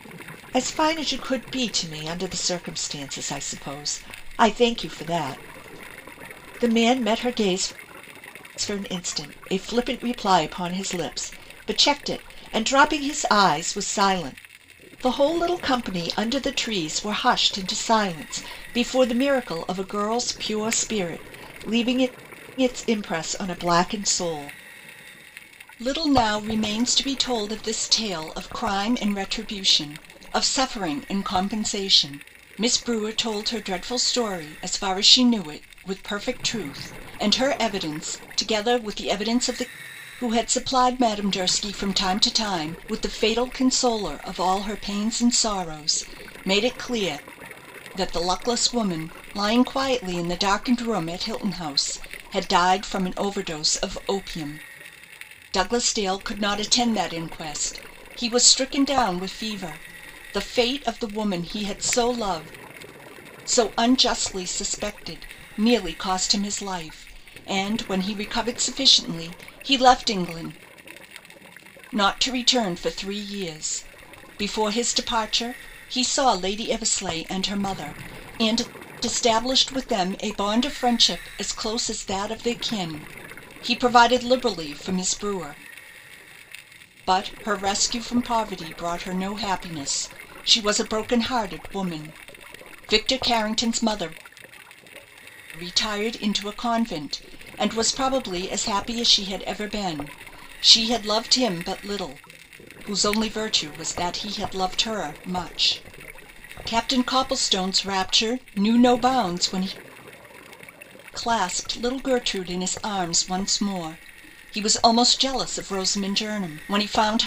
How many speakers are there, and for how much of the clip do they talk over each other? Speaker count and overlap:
one, no overlap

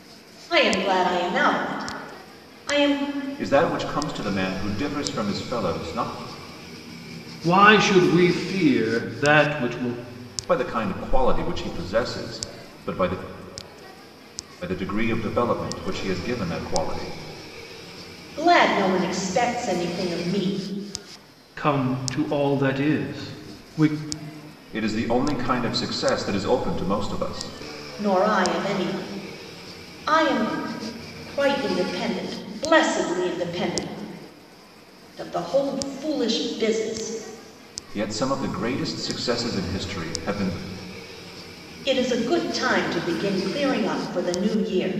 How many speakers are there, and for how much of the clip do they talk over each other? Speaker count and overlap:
three, no overlap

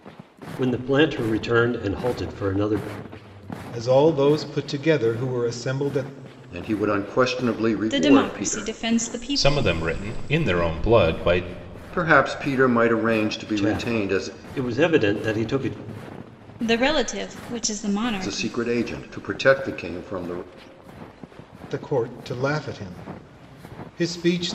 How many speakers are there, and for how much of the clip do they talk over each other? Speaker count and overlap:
five, about 10%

